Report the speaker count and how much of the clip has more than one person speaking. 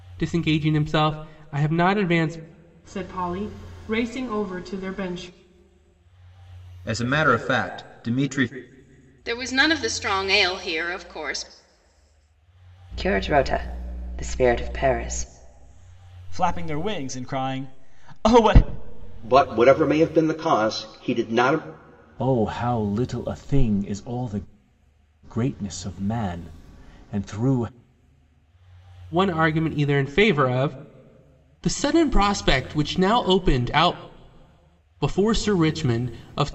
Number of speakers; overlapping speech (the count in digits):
8, no overlap